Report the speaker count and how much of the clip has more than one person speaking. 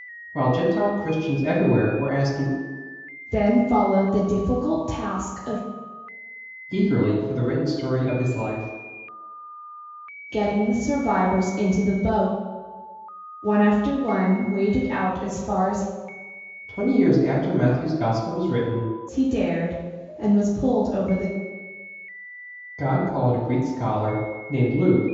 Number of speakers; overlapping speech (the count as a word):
two, no overlap